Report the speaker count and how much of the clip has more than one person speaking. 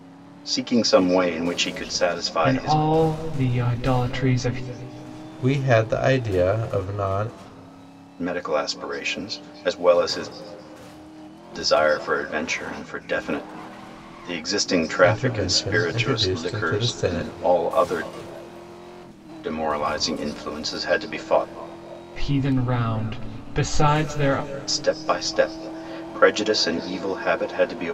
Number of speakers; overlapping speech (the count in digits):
3, about 10%